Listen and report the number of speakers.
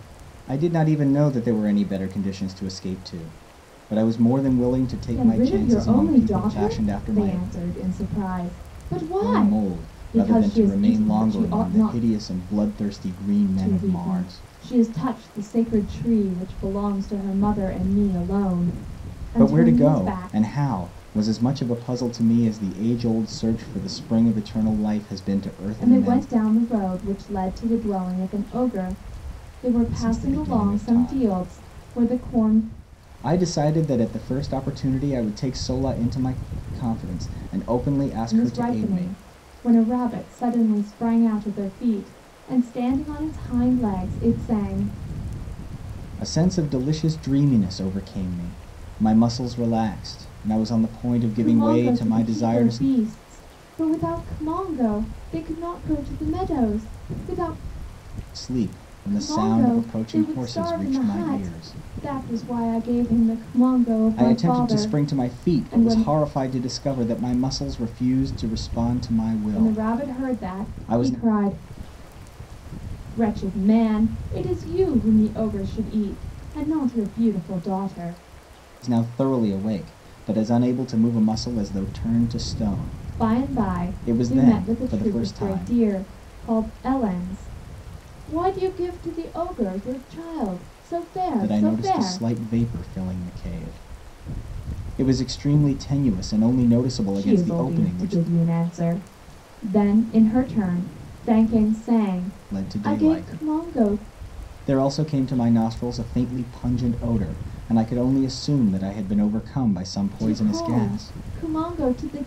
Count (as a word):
two